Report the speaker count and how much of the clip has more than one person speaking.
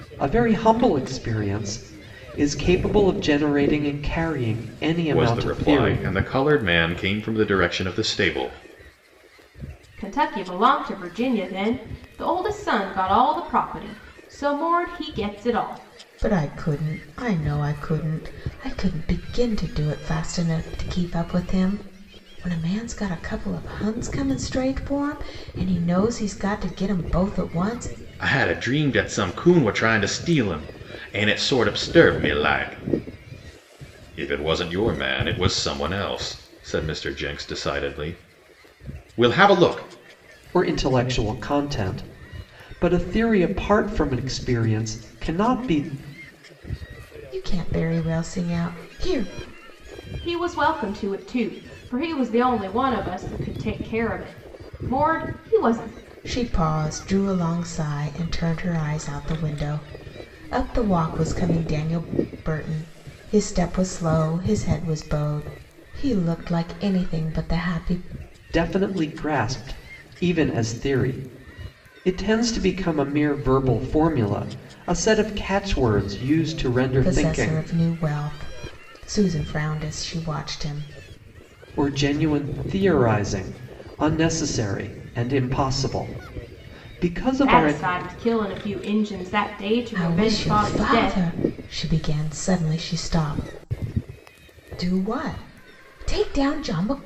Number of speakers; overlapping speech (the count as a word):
four, about 4%